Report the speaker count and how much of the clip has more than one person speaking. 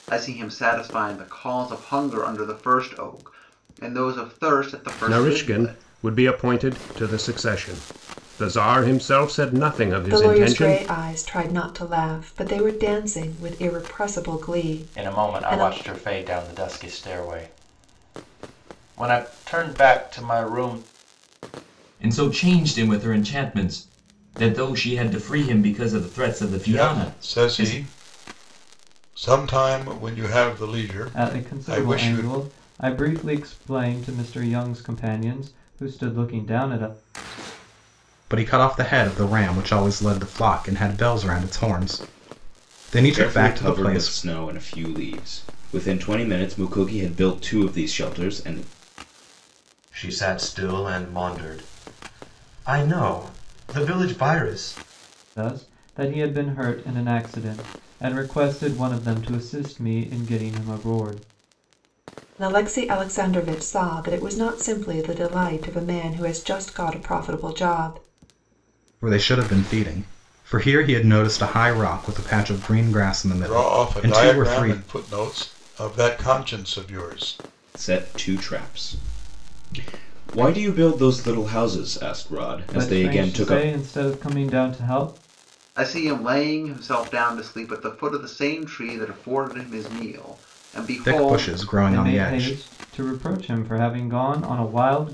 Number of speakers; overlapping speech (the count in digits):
10, about 10%